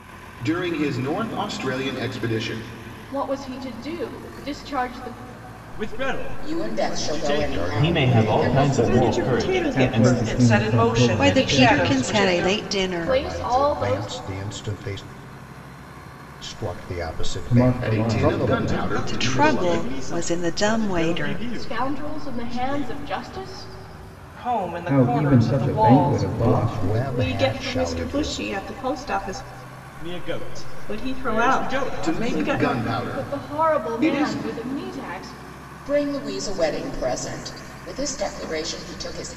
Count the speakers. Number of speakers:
ten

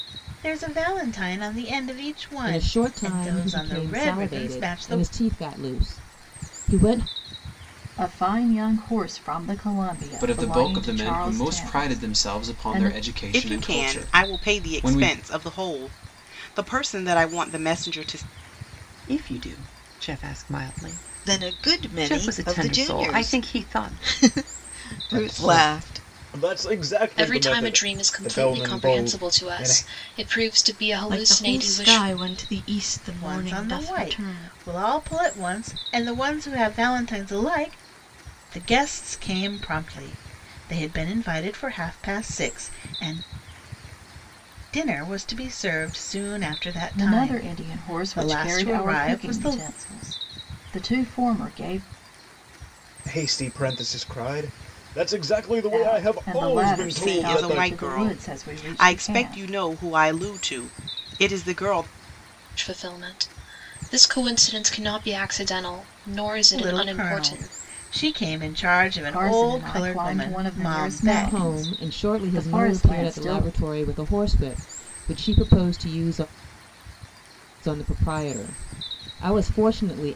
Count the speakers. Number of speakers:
ten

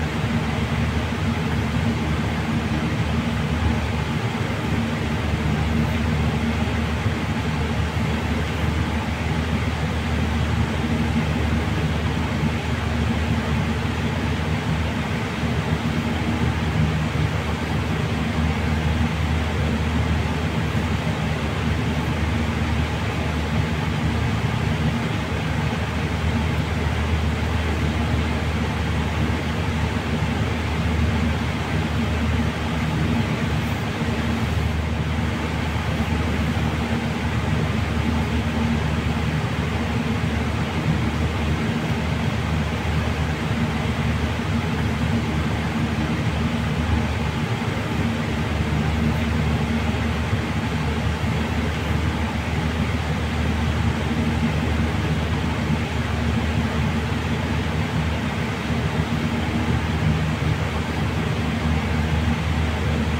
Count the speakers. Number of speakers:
zero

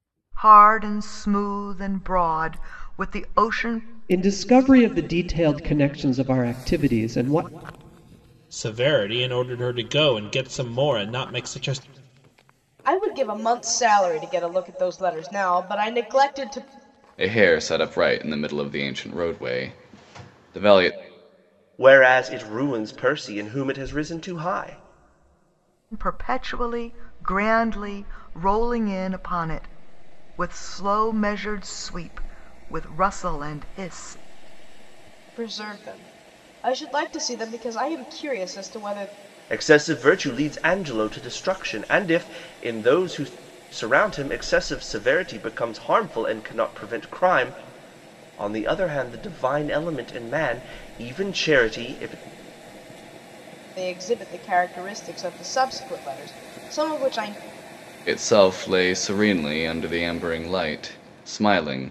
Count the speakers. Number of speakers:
six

